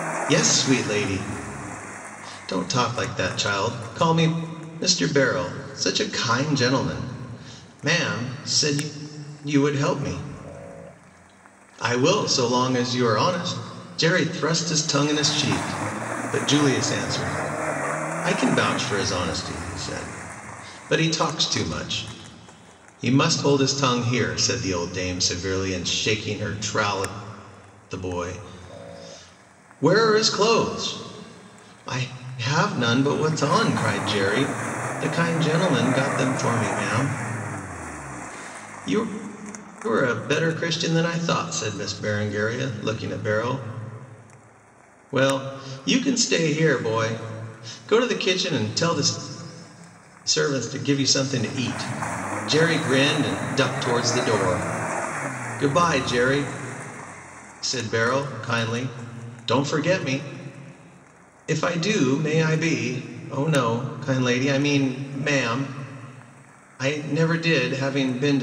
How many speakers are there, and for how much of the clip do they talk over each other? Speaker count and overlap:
one, no overlap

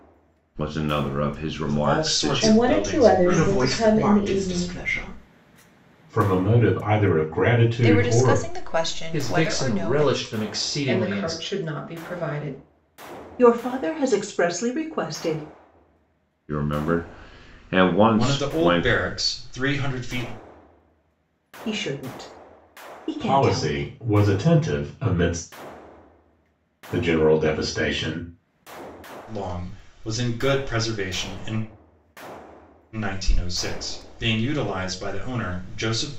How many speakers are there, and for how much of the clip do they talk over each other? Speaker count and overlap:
nine, about 20%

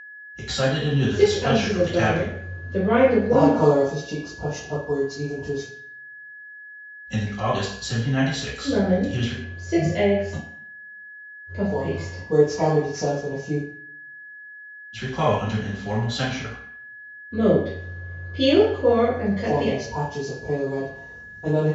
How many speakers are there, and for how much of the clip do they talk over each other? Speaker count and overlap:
three, about 15%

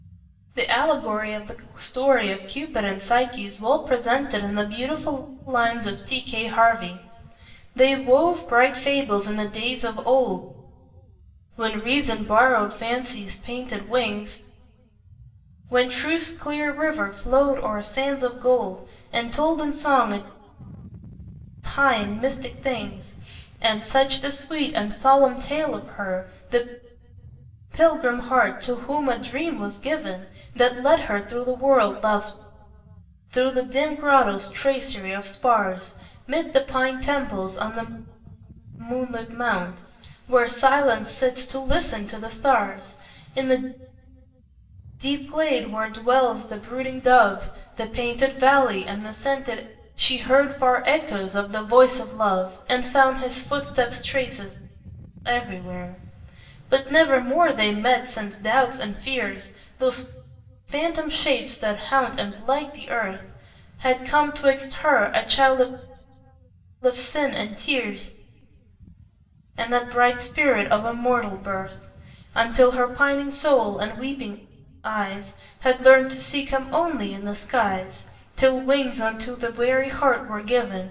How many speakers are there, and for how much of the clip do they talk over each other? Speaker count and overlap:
one, no overlap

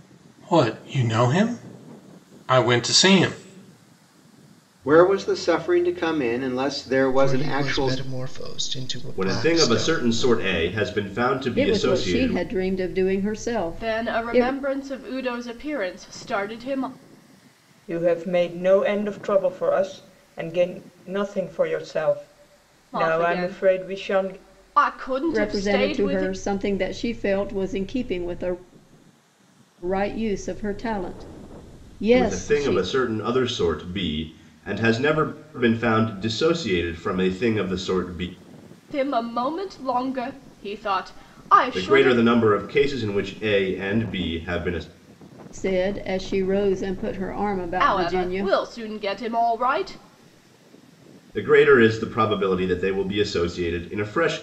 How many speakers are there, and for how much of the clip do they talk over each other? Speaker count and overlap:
seven, about 15%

